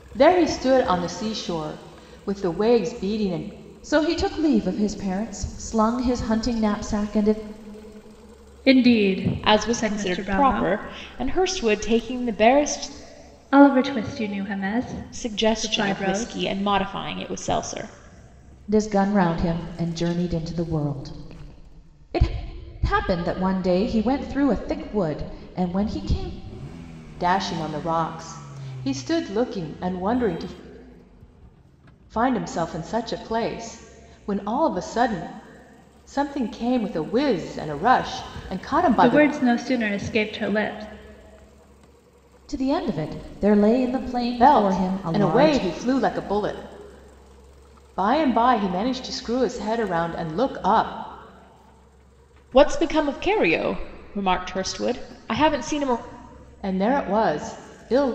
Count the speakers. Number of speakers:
4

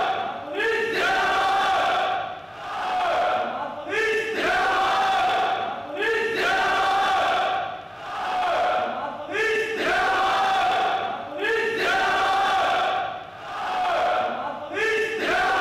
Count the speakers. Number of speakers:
0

